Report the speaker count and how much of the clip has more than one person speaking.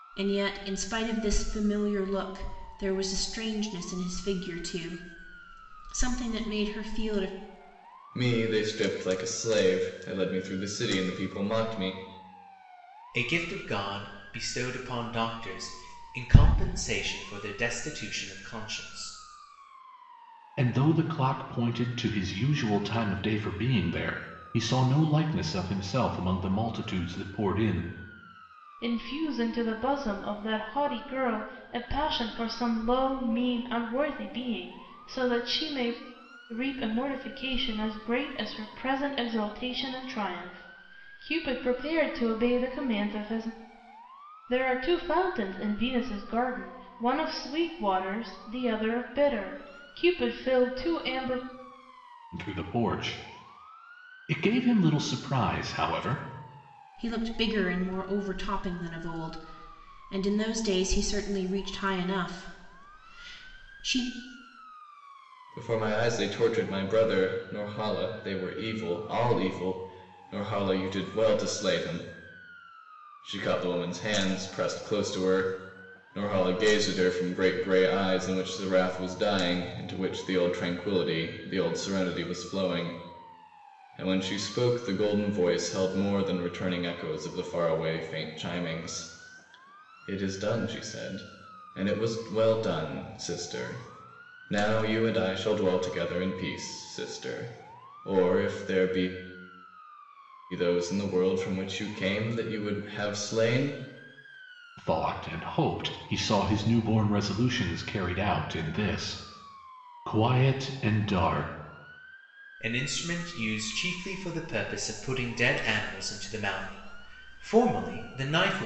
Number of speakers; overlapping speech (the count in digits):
5, no overlap